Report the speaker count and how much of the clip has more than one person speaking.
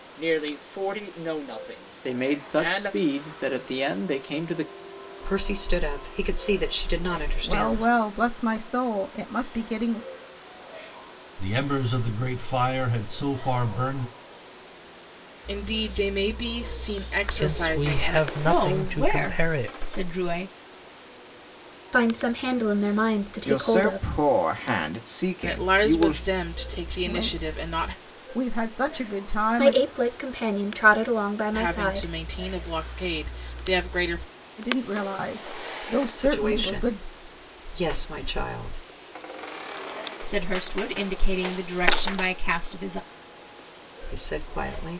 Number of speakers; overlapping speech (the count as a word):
ten, about 18%